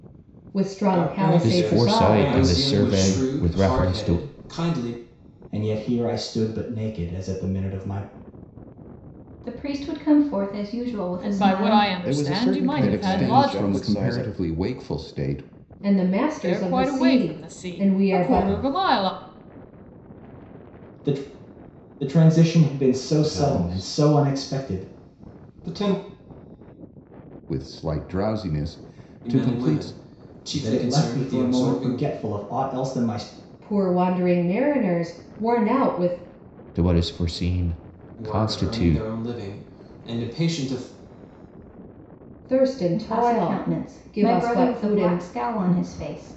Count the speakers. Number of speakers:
9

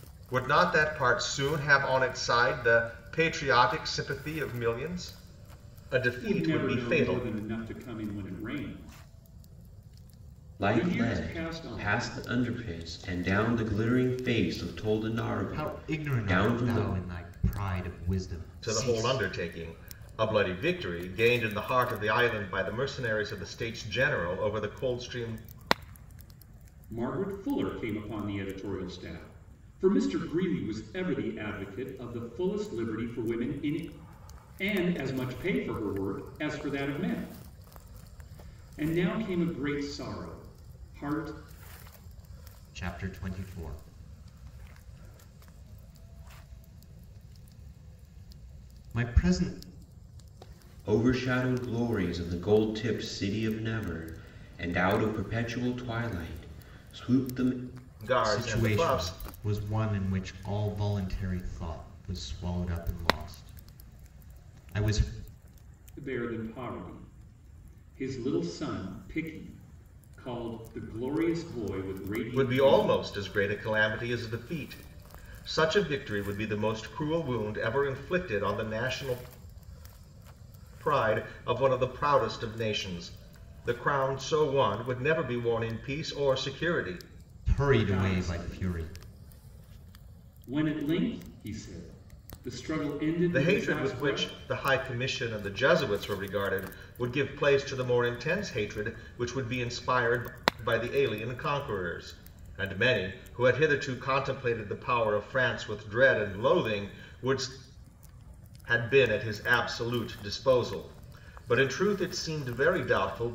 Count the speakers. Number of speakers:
4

